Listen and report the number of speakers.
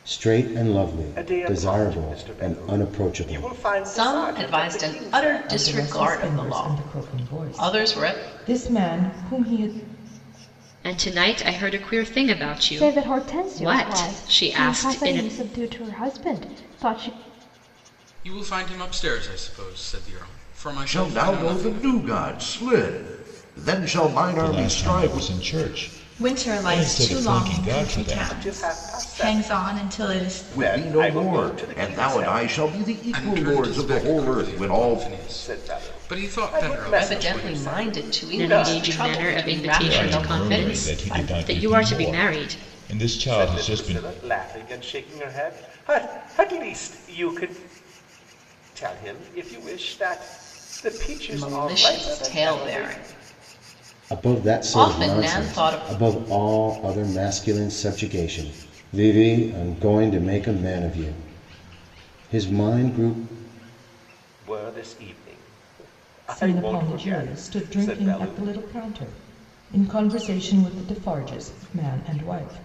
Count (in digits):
10